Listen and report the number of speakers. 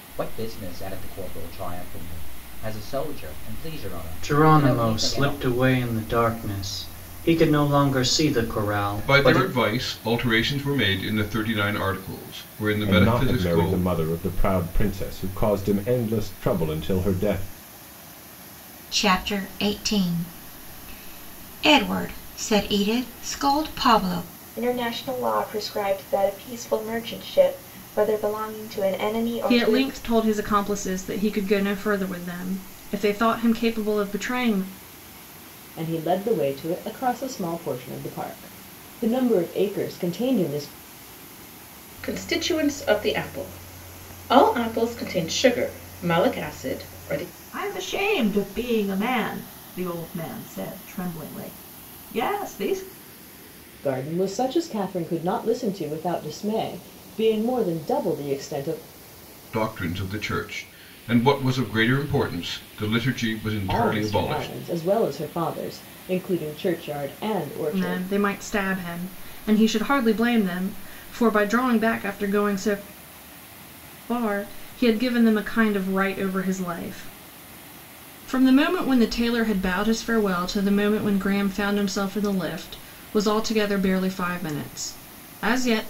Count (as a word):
ten